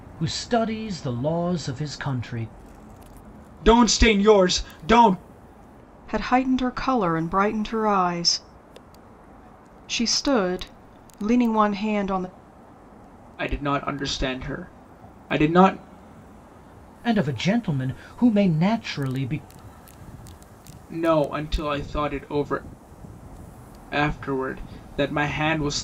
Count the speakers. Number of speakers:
3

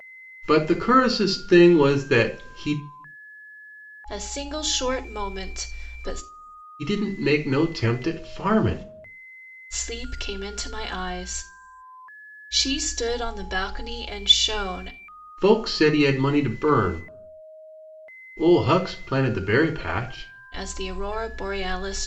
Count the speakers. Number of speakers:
2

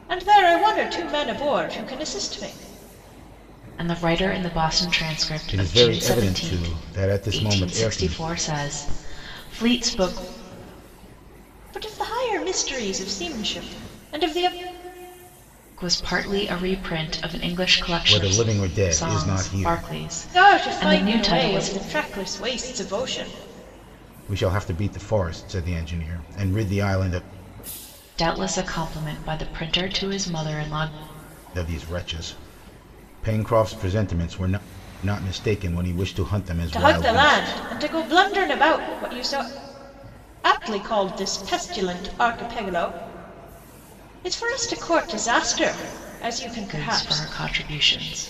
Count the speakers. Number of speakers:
3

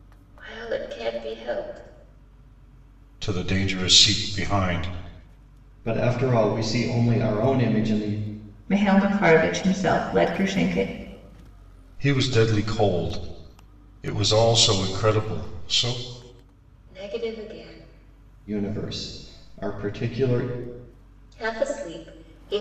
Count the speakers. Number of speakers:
4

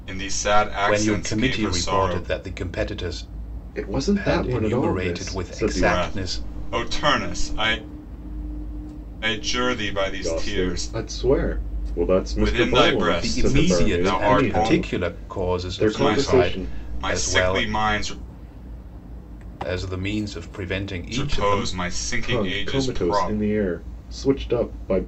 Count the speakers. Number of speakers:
3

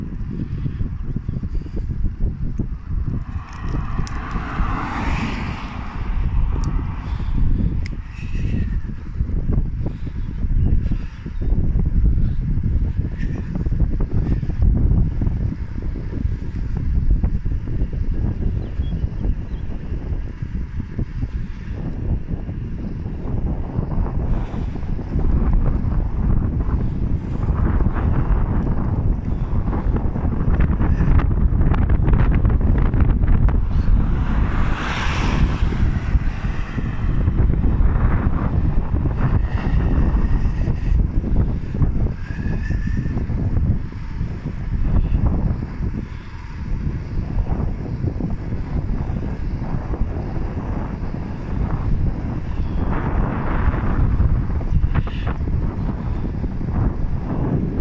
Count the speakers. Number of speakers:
0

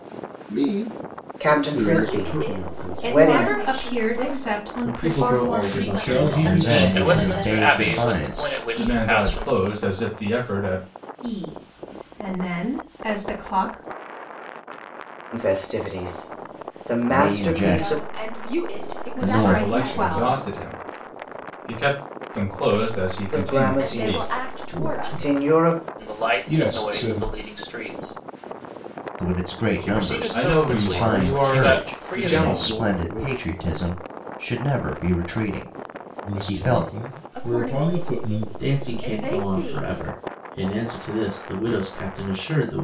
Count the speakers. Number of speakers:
10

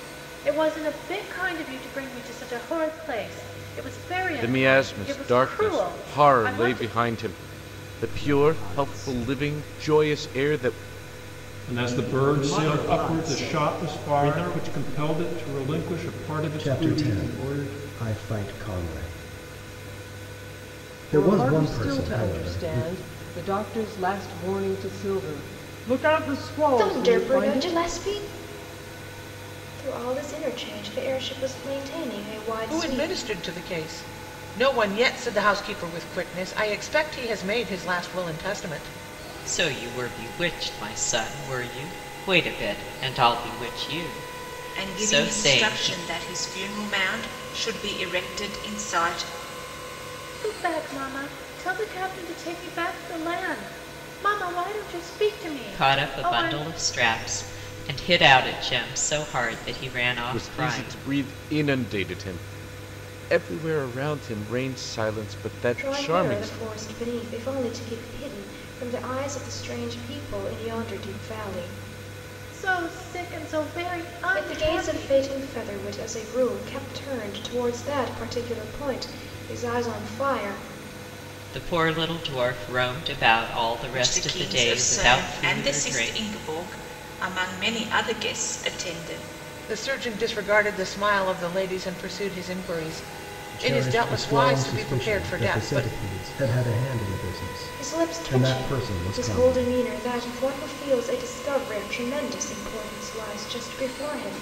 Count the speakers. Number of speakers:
10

